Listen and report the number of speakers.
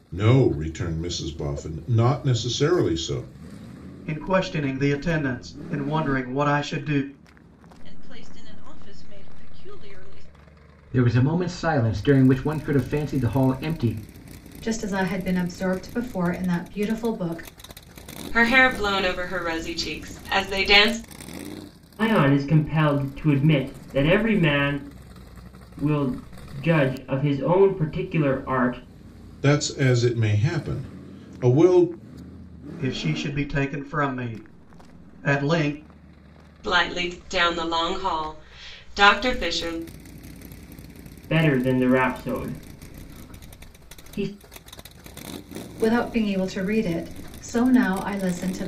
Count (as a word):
seven